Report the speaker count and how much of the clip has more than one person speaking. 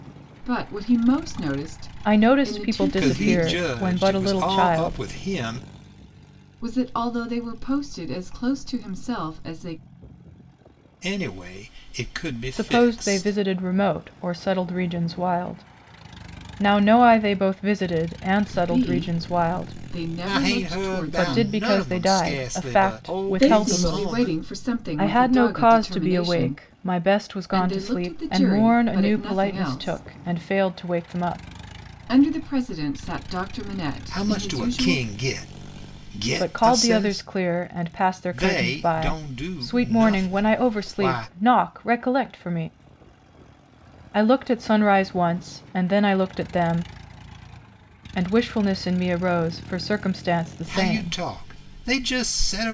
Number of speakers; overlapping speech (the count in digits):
3, about 35%